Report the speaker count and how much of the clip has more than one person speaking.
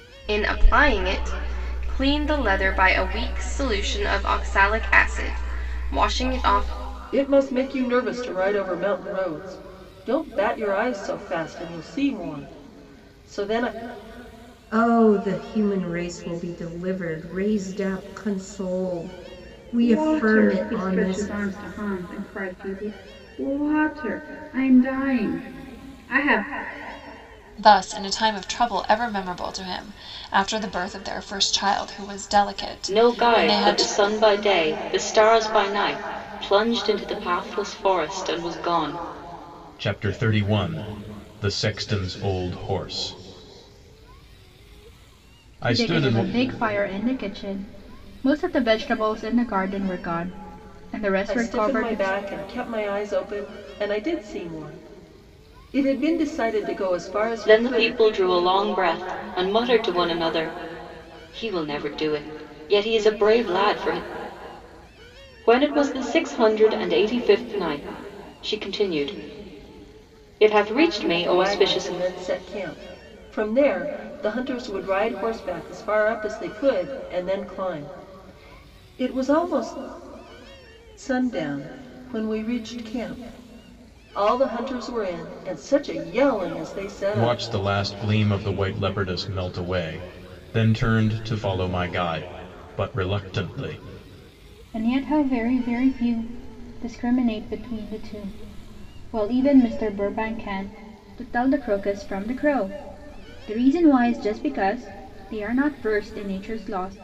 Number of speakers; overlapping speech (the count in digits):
8, about 5%